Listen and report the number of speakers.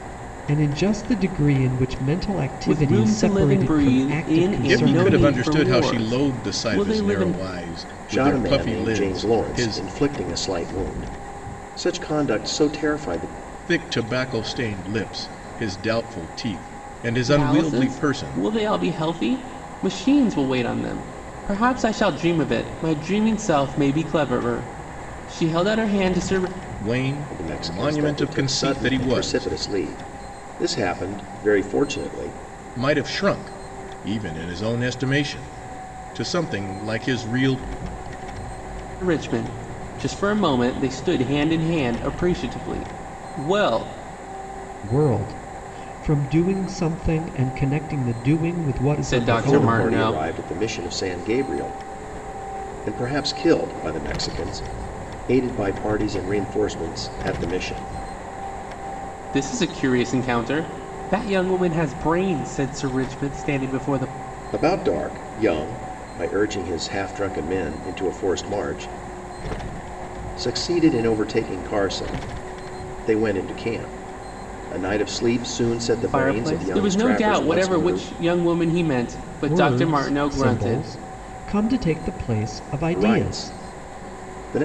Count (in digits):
4